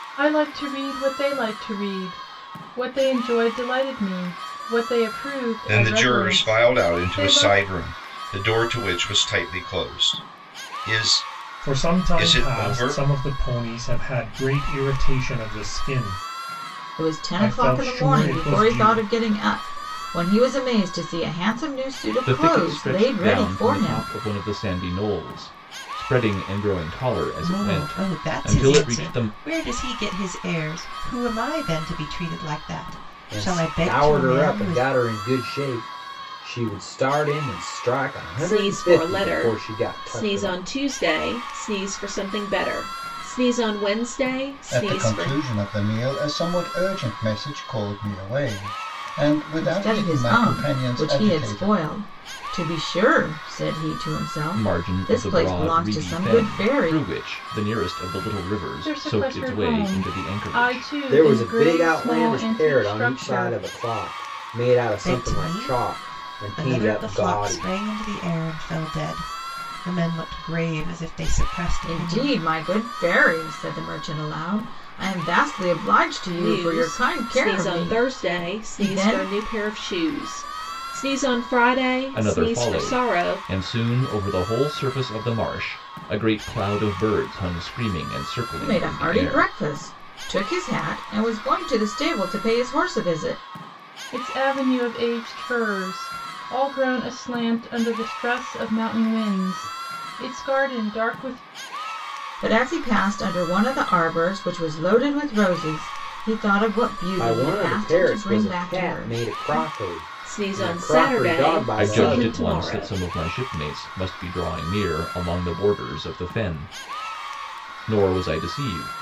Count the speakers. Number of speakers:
9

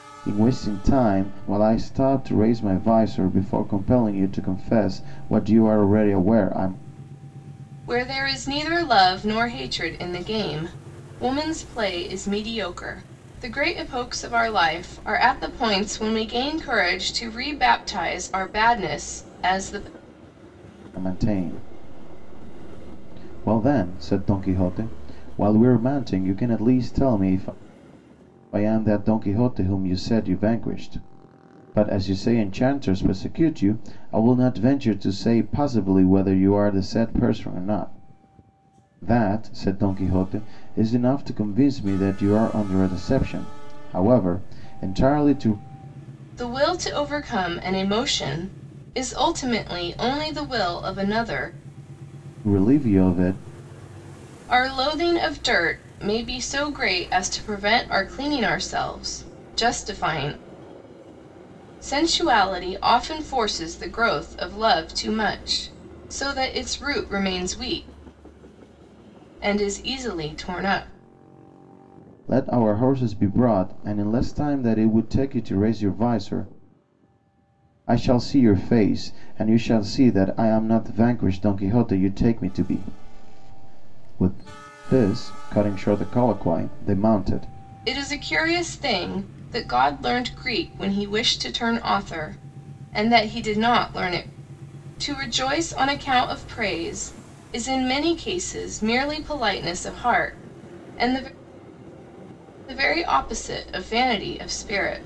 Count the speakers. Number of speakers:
2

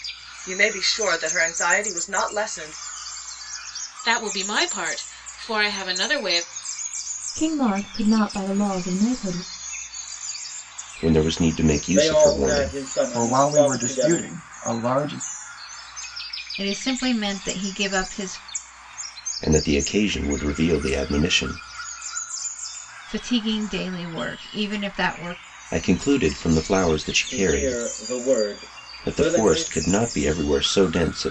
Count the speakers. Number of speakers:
7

